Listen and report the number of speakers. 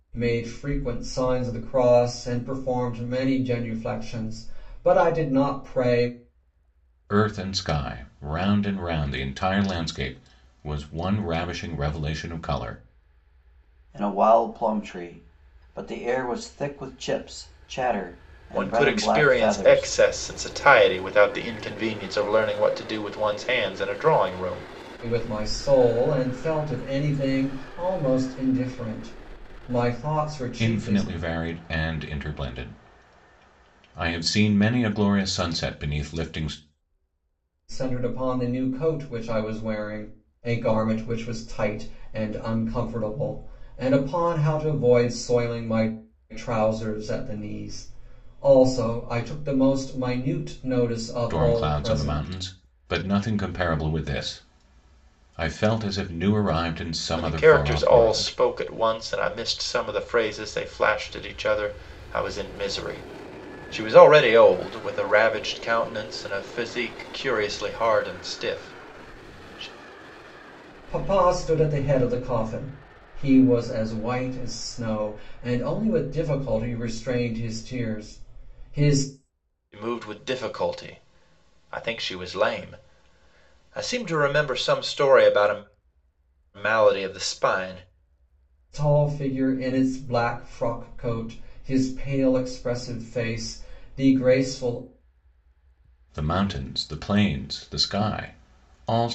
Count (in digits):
4